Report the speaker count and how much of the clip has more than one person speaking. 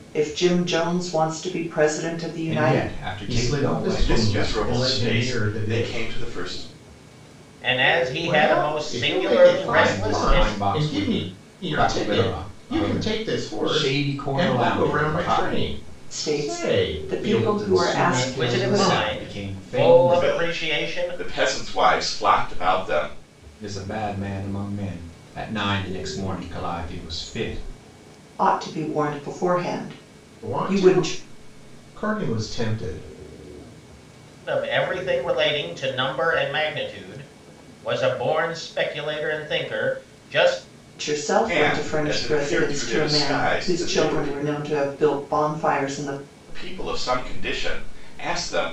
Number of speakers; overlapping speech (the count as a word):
five, about 38%